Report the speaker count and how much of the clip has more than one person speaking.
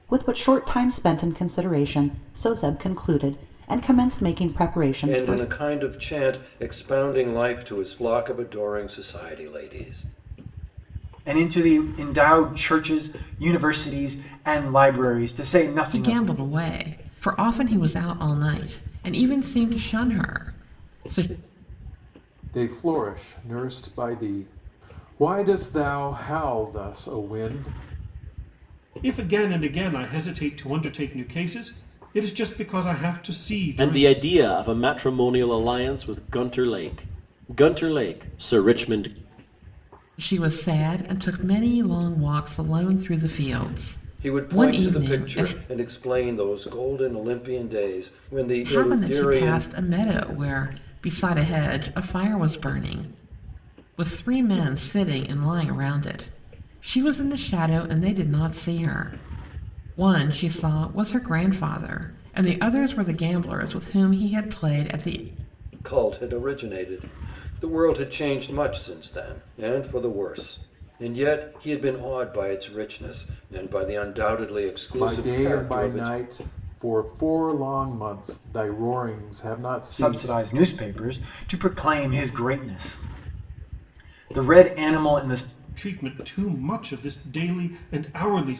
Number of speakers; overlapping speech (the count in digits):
7, about 6%